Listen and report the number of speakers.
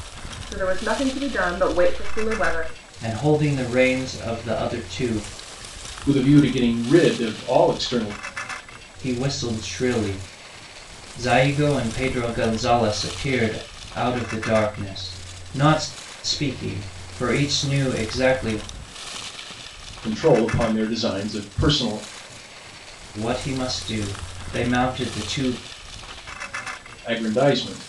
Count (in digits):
3